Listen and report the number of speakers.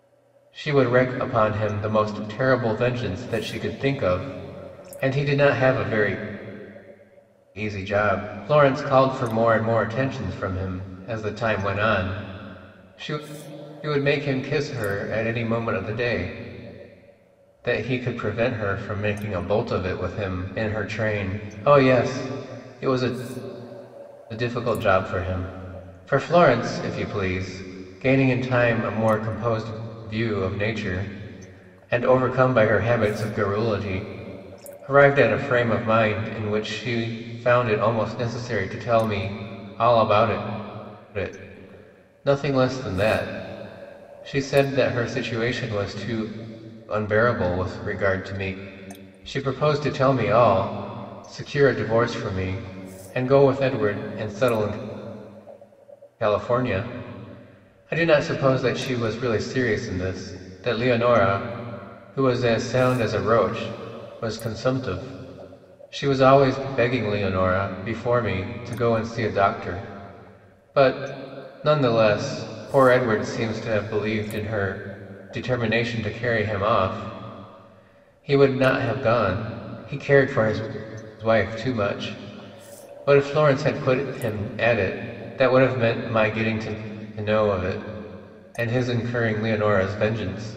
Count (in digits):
1